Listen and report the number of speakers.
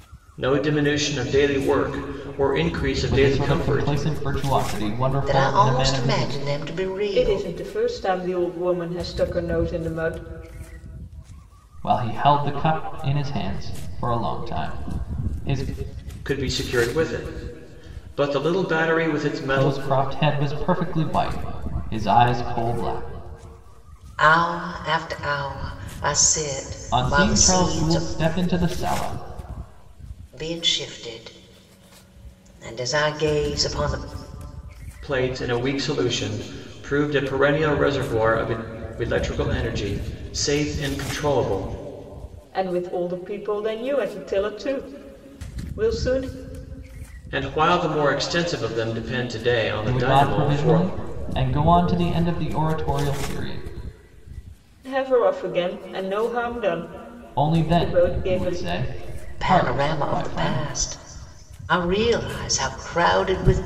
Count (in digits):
4